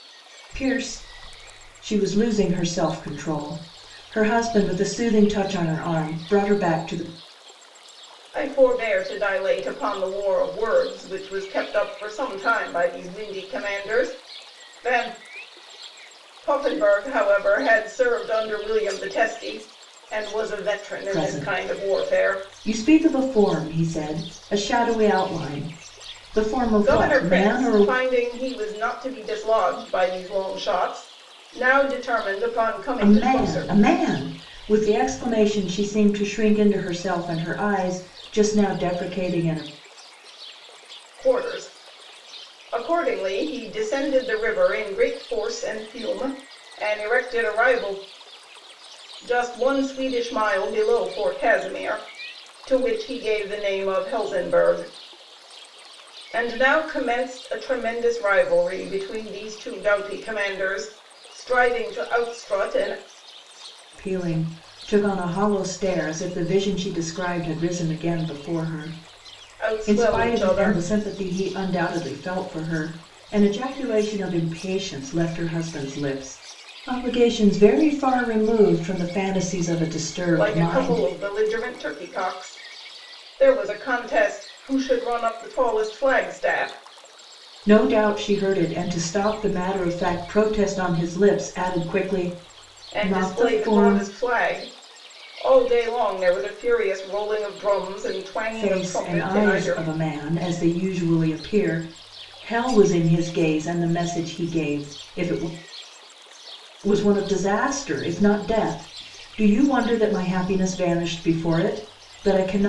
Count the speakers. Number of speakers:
2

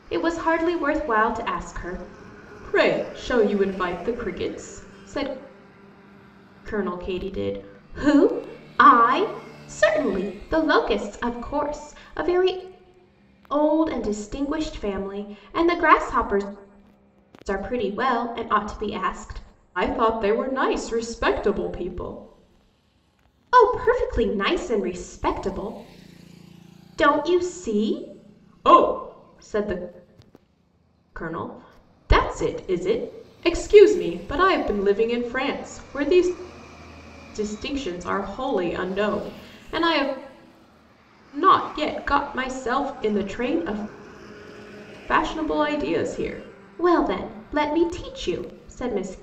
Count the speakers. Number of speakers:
1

